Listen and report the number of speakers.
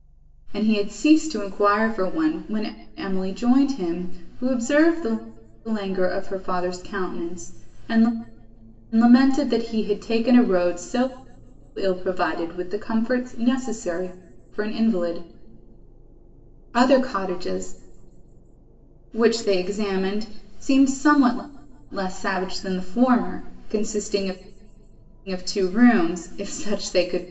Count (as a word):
one